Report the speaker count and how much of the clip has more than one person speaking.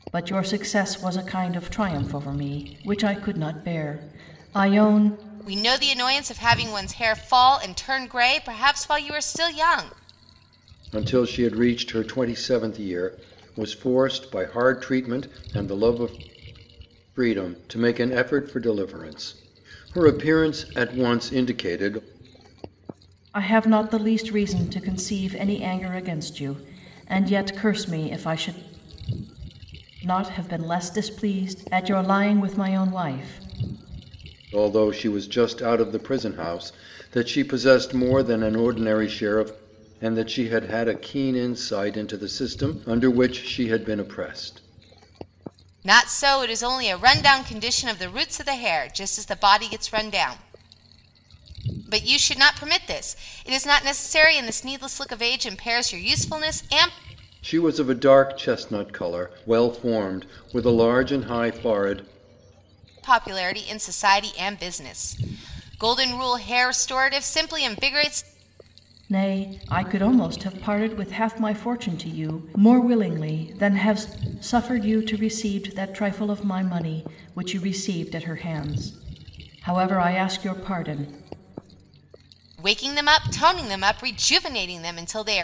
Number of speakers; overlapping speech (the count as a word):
three, no overlap